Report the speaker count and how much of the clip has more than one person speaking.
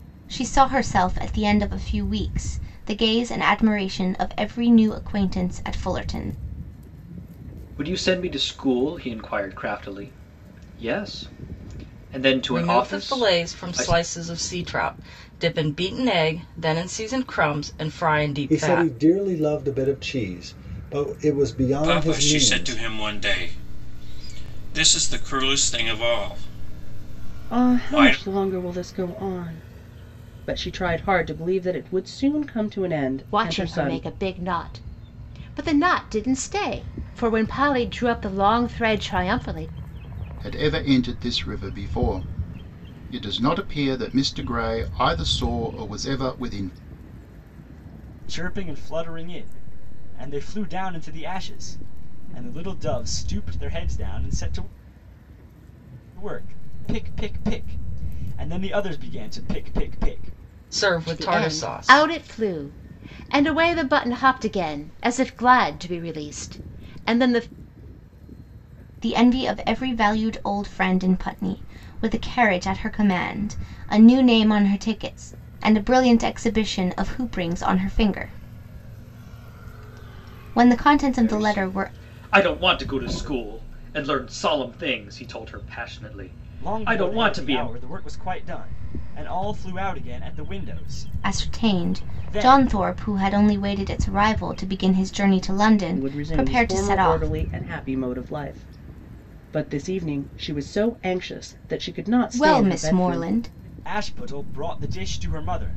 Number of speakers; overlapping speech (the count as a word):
nine, about 11%